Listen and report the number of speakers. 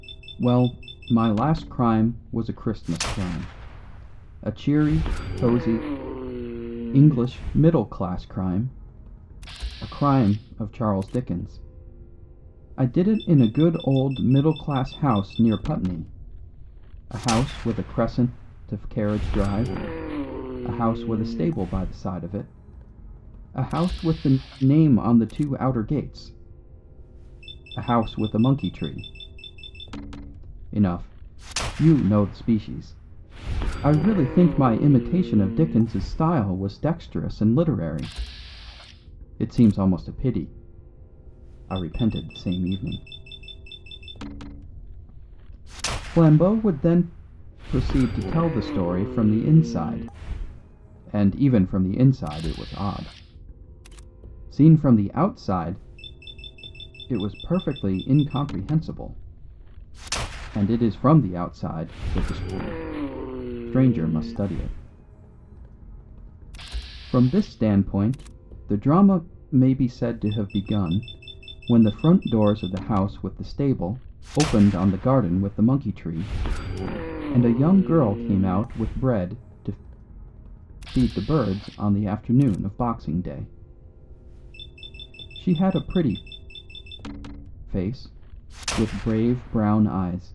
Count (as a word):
one